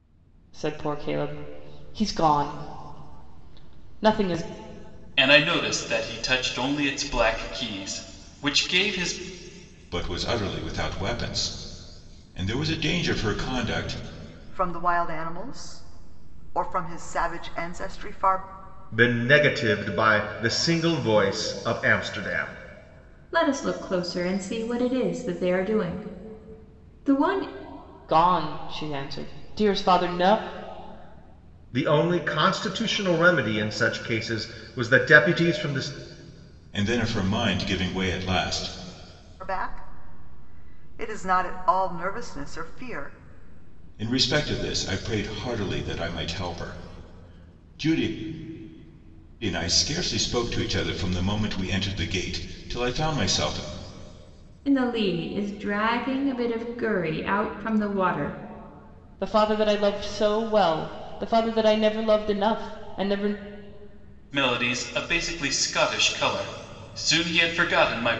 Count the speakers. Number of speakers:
6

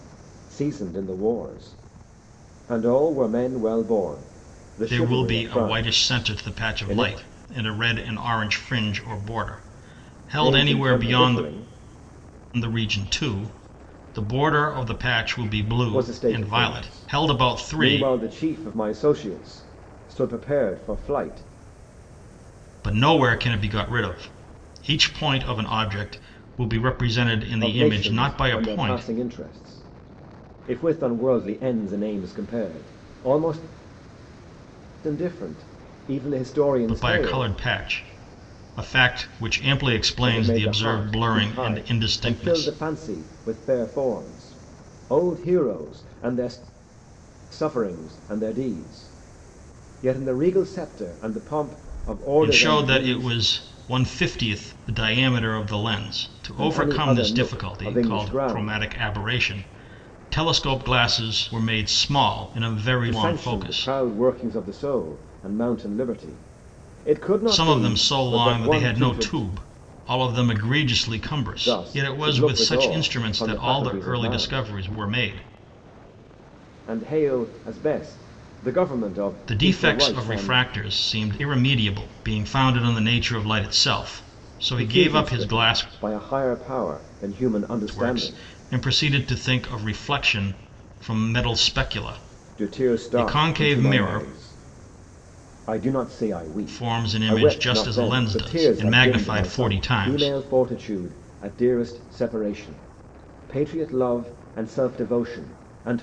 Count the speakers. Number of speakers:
2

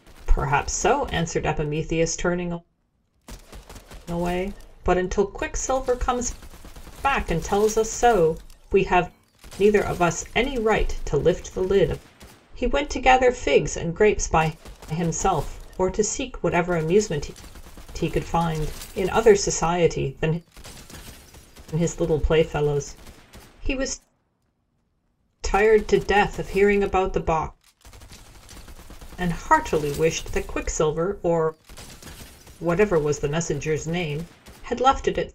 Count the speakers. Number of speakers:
1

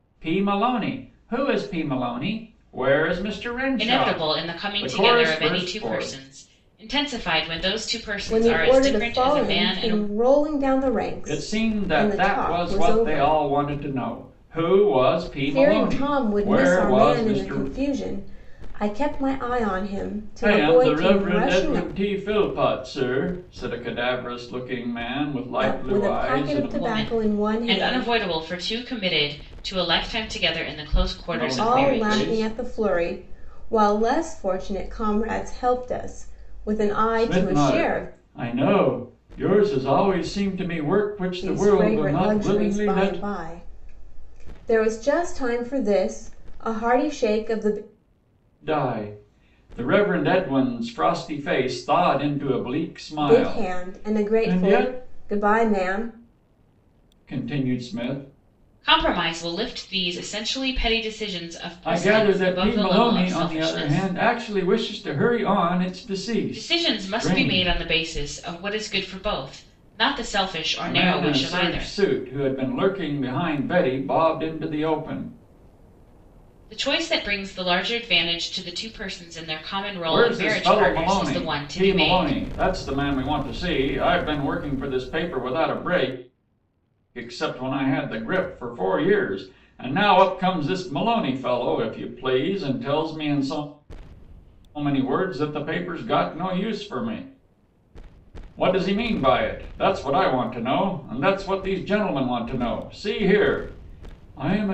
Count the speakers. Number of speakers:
3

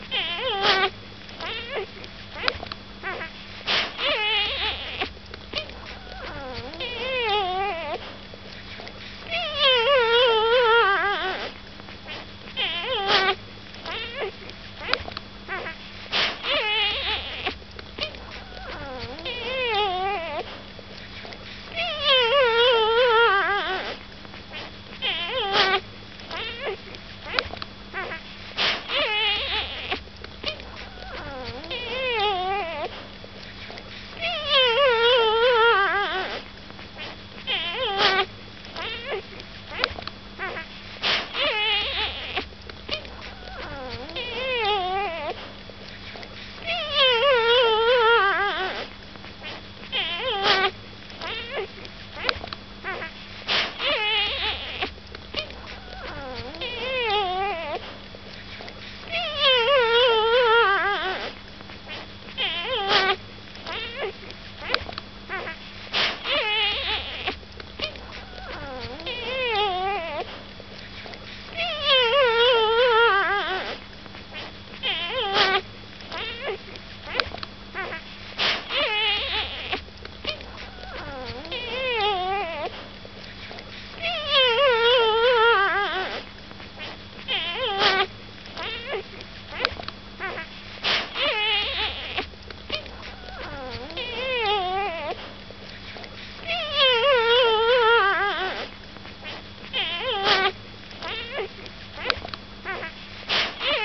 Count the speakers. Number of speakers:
0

